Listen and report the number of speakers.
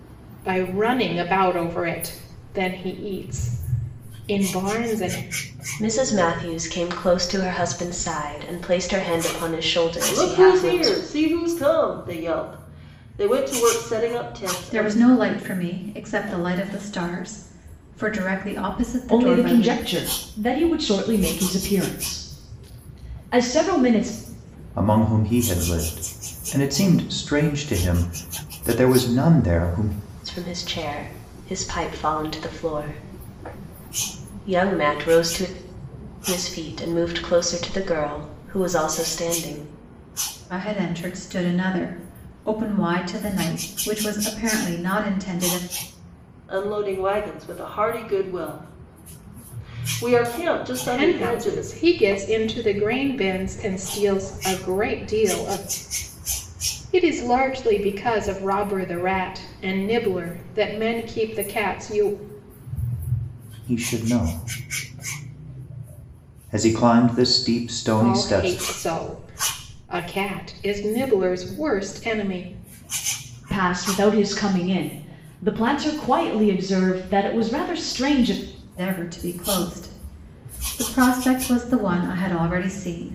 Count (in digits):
6